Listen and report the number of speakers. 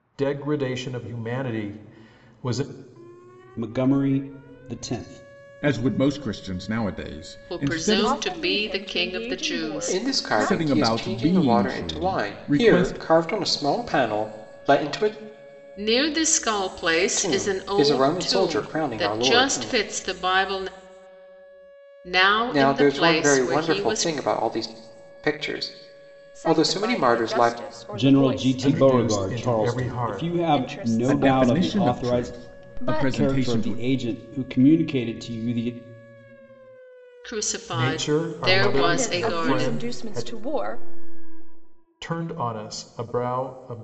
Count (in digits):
6